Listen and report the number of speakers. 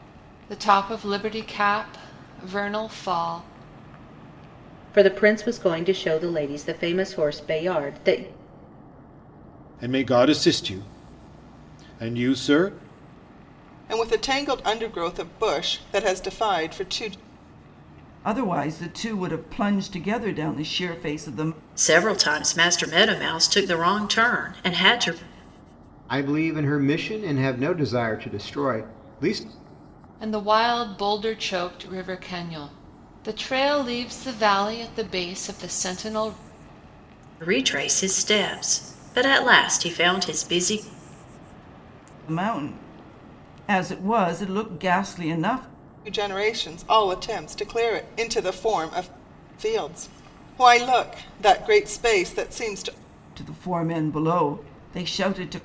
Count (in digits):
7